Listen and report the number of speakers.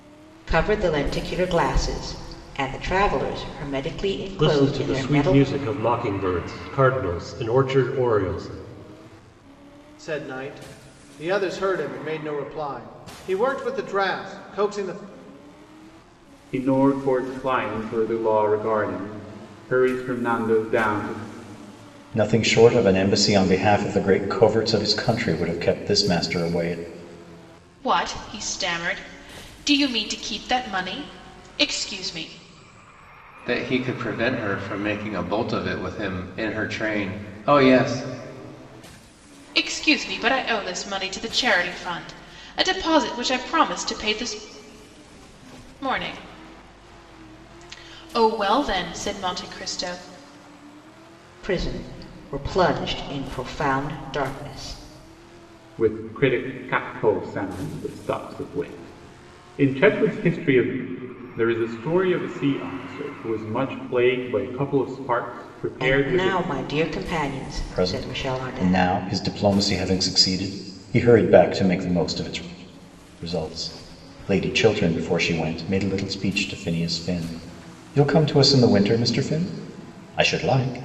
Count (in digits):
7